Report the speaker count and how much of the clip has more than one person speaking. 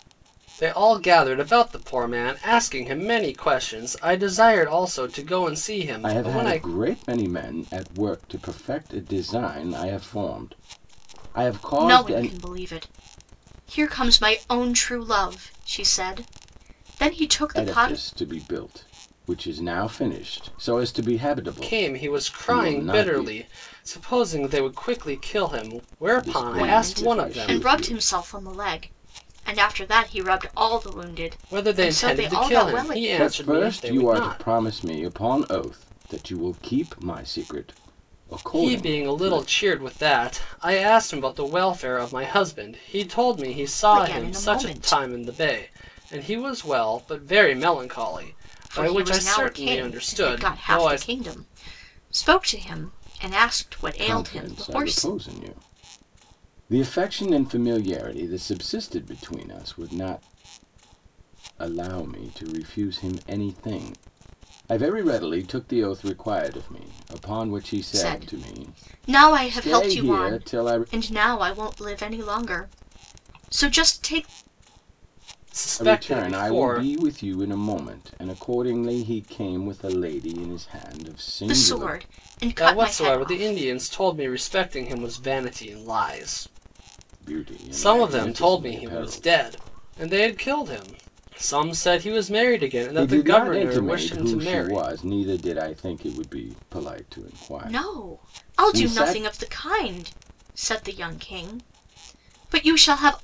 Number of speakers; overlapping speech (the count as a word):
three, about 24%